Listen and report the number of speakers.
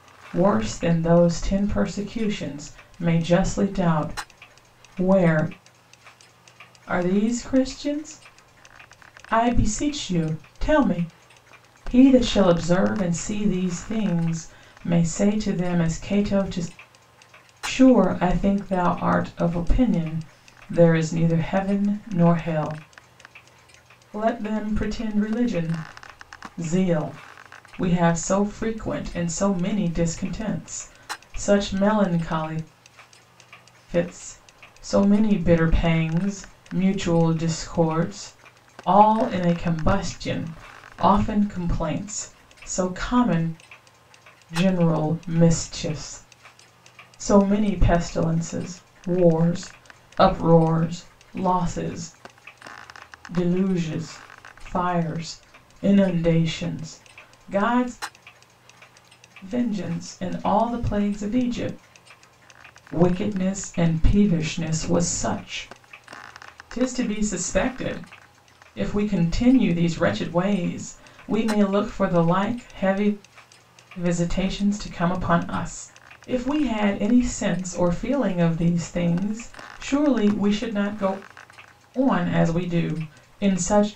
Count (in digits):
1